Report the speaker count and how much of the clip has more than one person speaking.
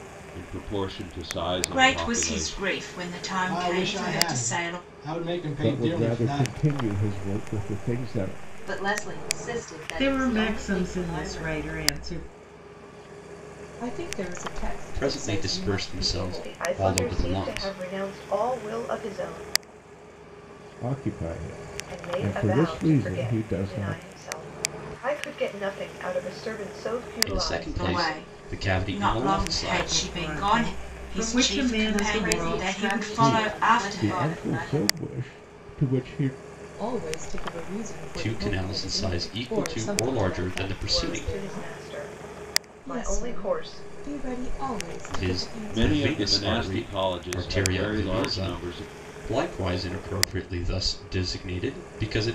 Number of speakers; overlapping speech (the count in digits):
10, about 55%